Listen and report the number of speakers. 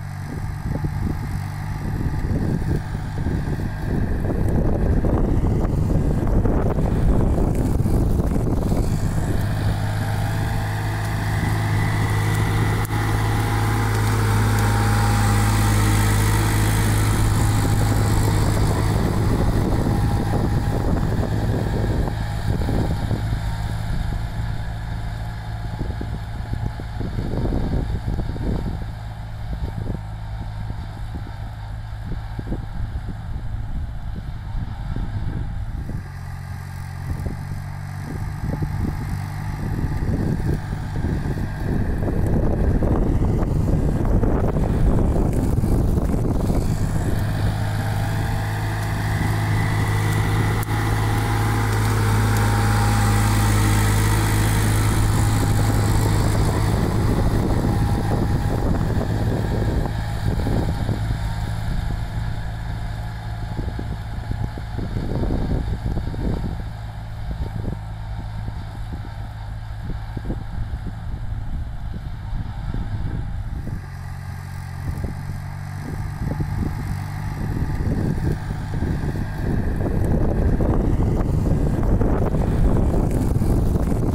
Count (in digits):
0